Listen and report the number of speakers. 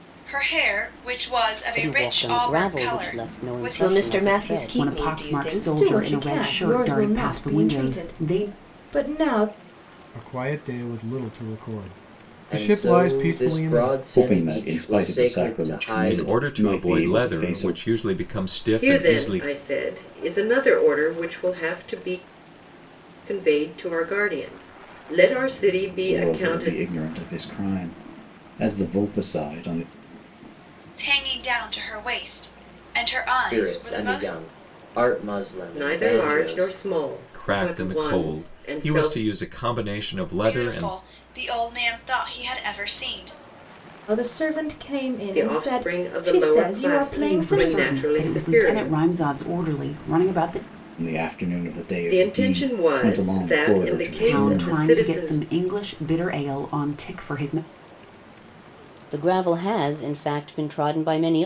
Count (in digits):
10